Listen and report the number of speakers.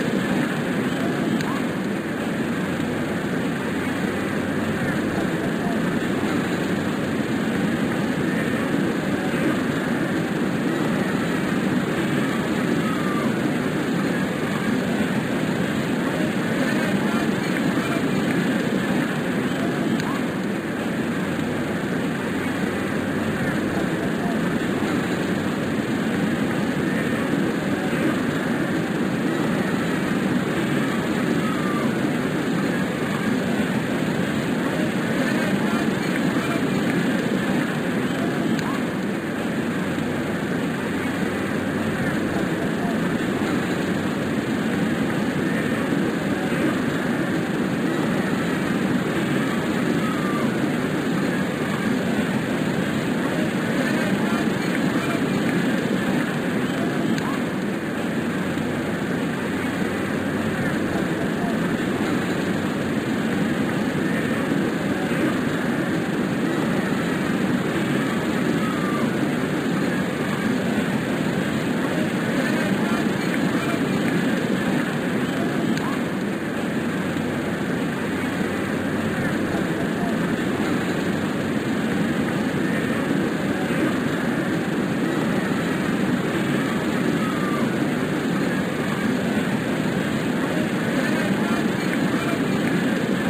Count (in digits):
0